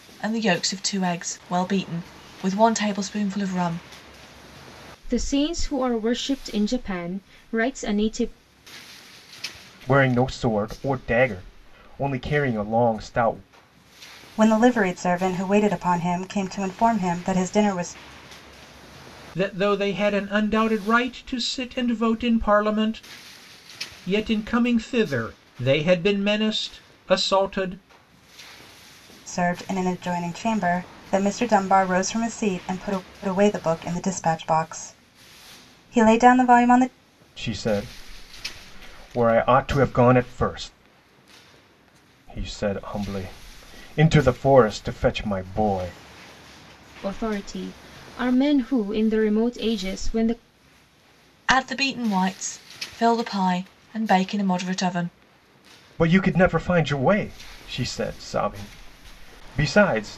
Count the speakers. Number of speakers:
five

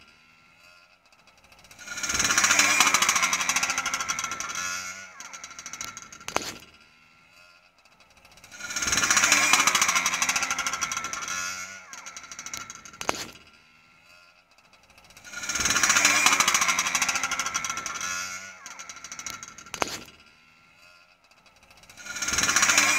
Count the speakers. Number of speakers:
zero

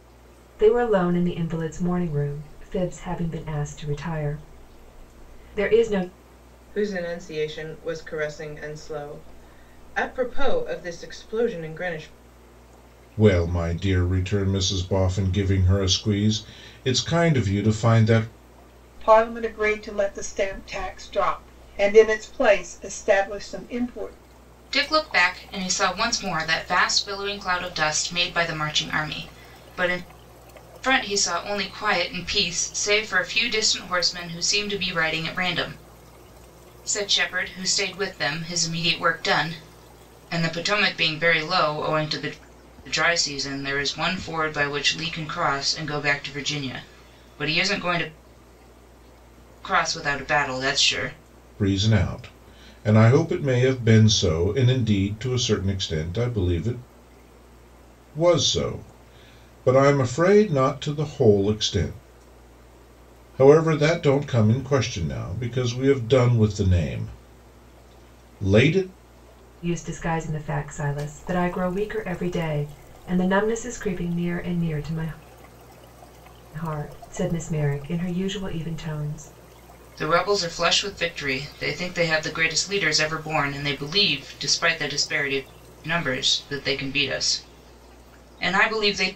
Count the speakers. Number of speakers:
five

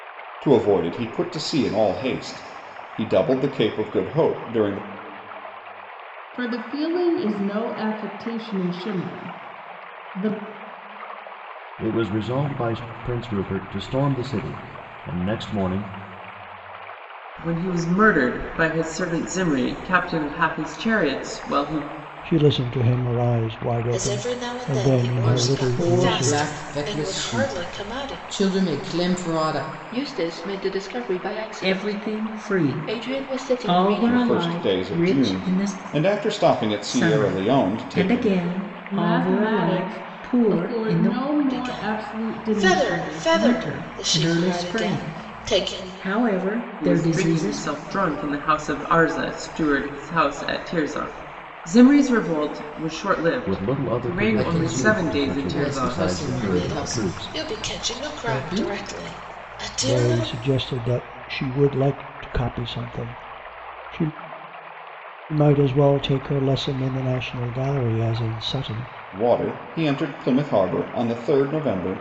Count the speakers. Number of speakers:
nine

